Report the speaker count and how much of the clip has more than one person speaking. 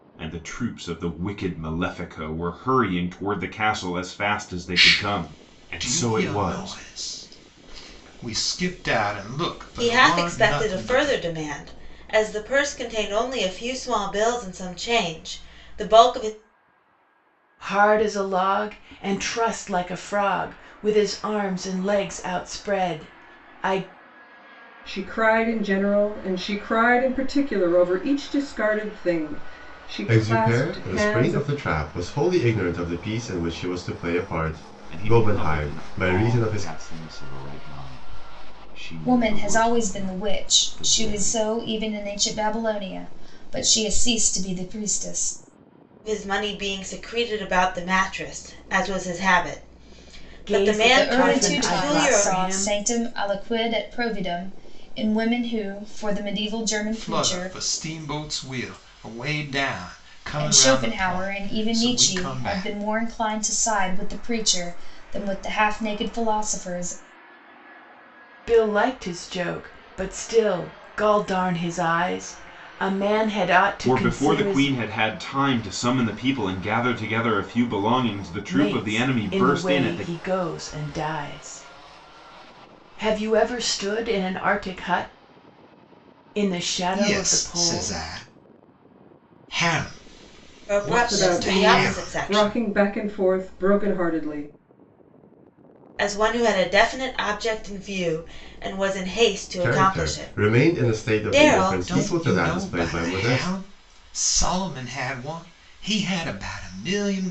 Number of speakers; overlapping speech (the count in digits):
8, about 23%